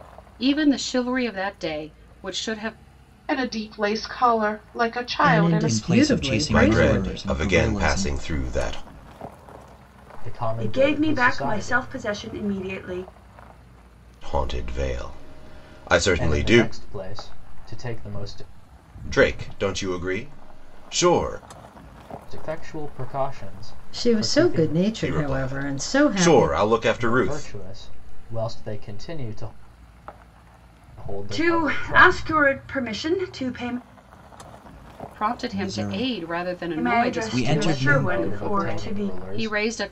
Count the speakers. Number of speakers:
seven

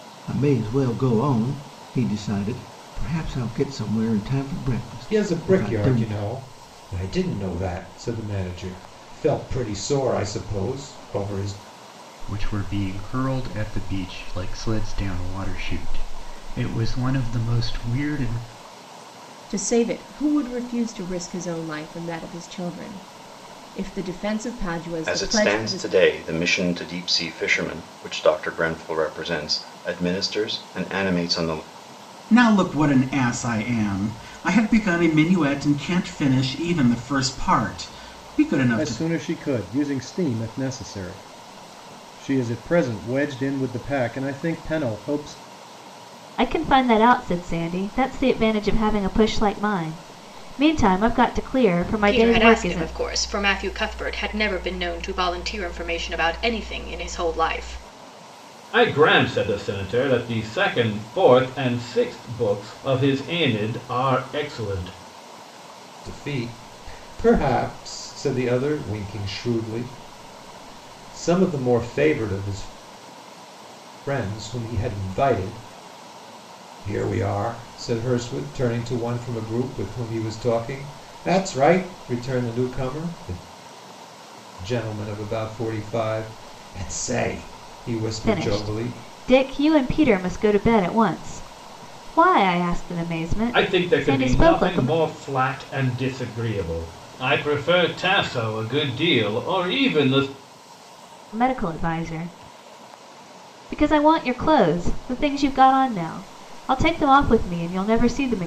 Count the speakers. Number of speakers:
ten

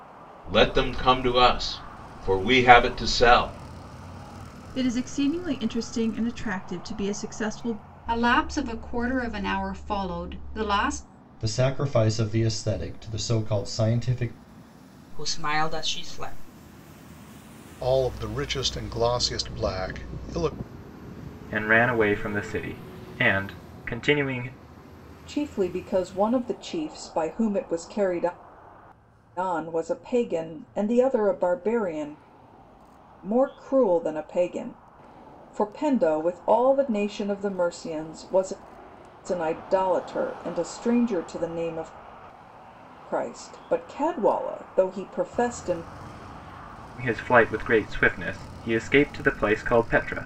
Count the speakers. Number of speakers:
eight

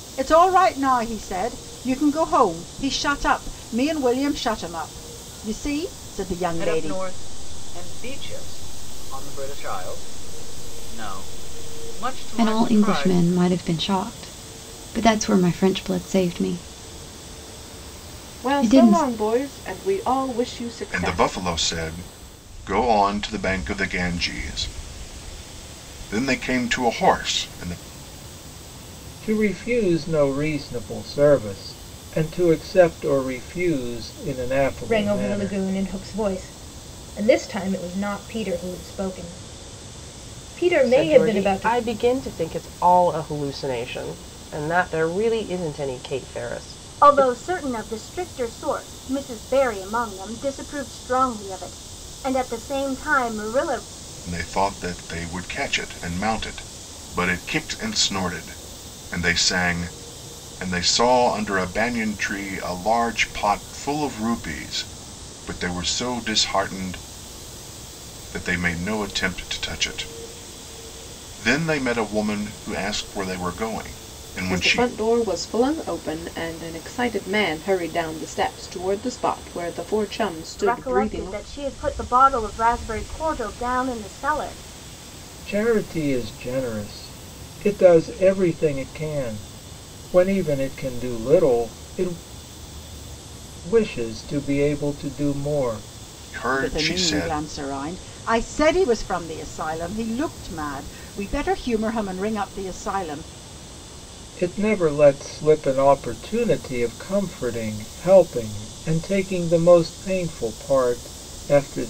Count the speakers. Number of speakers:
nine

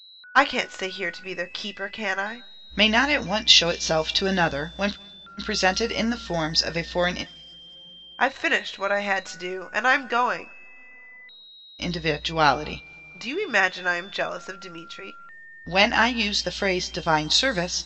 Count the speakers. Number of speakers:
two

